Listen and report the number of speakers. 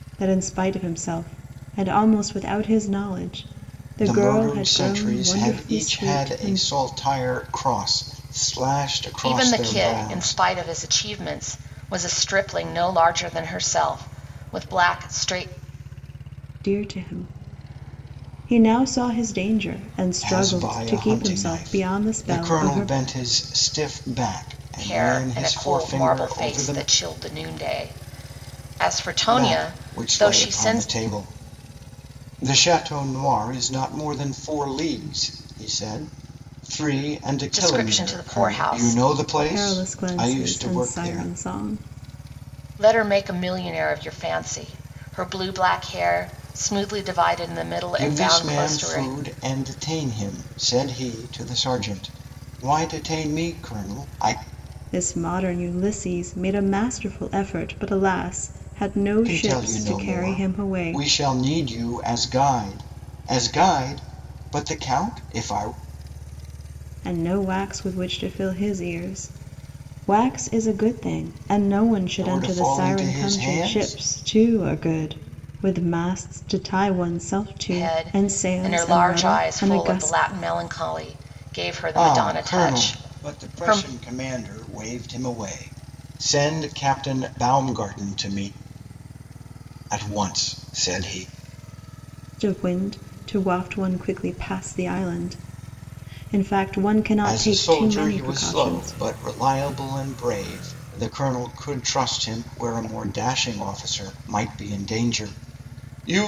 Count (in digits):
3